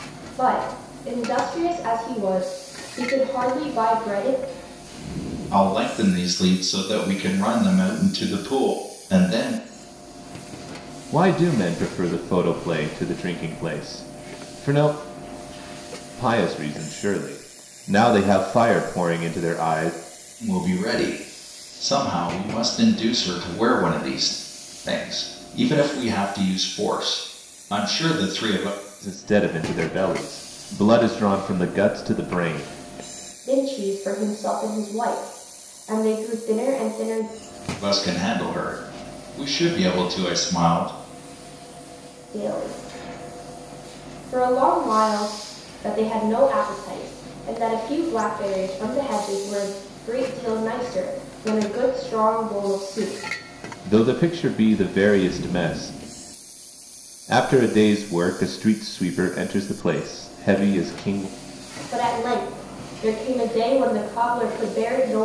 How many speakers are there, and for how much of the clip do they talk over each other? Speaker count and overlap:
3, no overlap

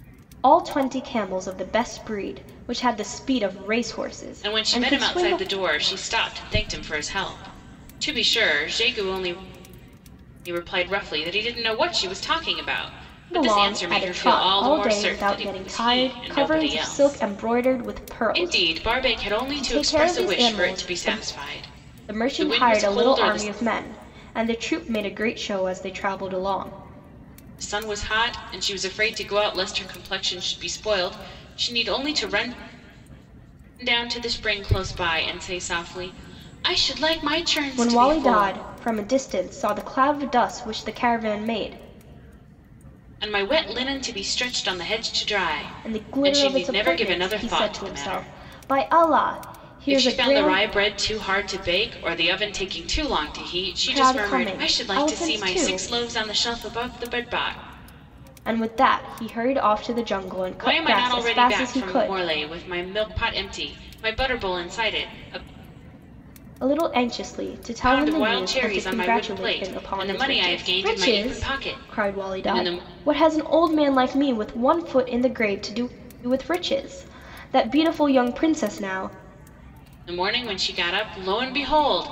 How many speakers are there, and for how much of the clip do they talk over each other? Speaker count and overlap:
2, about 27%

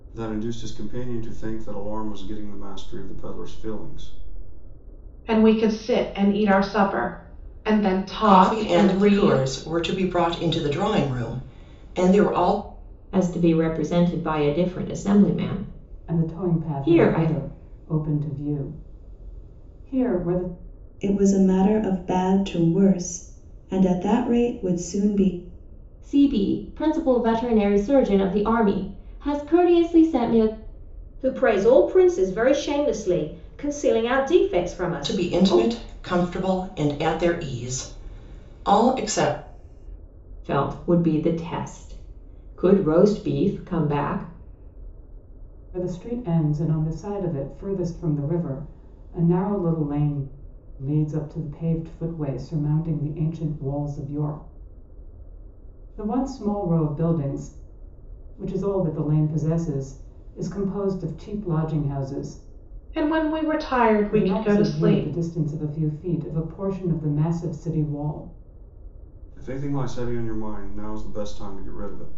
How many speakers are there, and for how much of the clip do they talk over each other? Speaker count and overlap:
8, about 6%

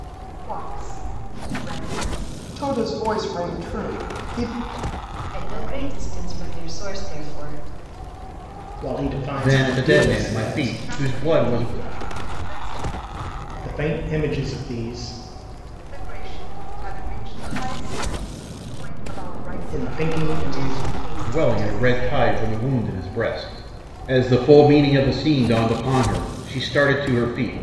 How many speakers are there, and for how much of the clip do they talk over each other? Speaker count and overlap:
5, about 18%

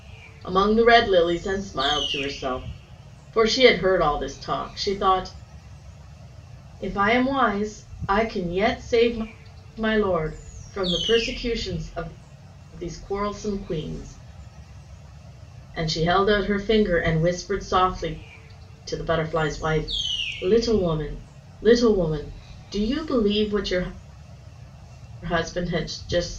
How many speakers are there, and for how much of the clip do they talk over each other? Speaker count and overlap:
1, no overlap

